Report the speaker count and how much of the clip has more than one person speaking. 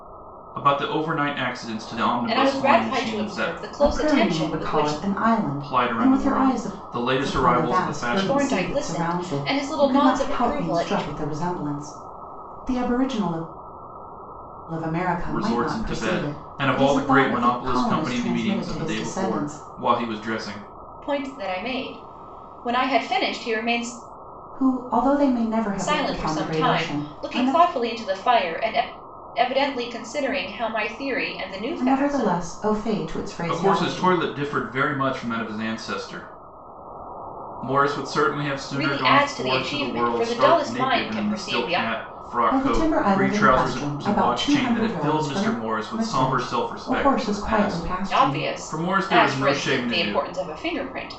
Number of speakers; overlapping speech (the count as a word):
three, about 50%